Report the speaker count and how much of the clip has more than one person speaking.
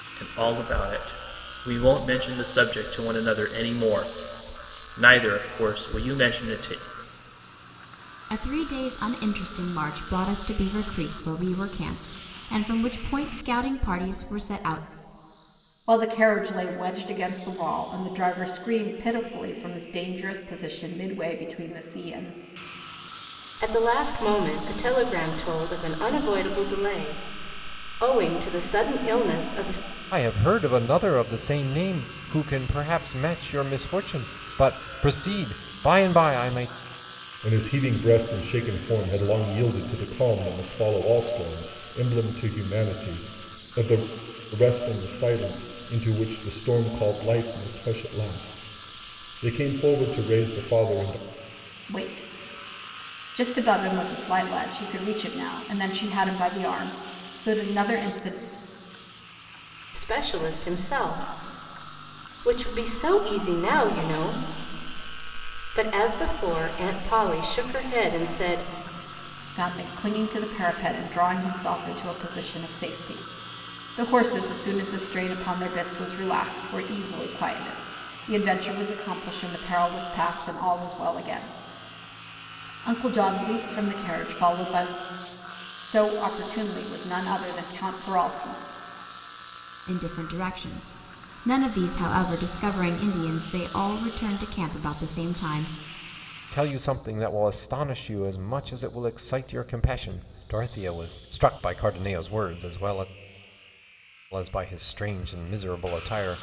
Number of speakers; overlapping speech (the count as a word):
six, no overlap